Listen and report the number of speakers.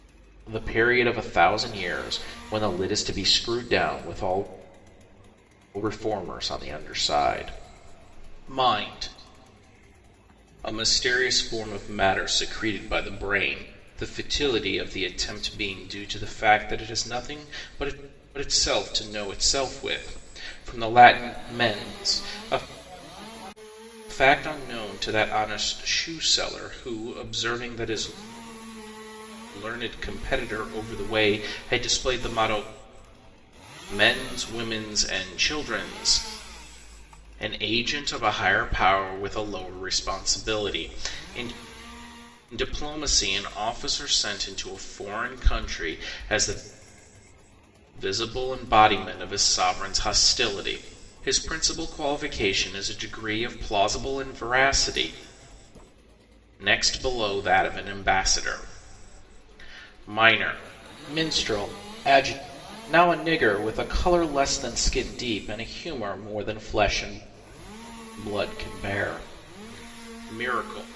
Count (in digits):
1